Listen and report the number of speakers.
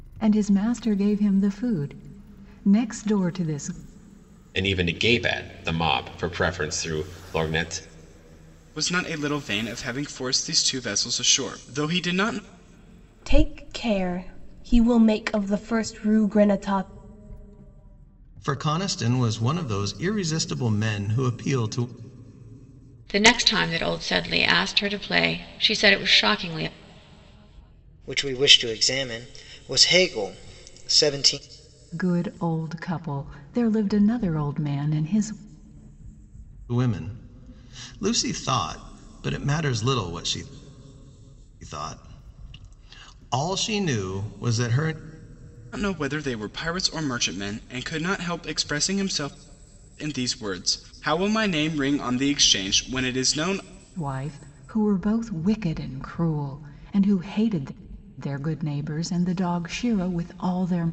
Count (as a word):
seven